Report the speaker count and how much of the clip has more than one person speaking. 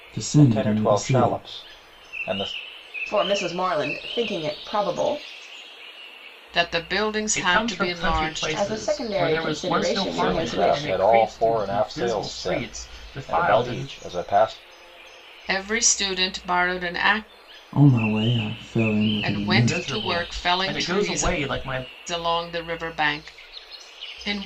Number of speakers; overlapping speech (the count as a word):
five, about 40%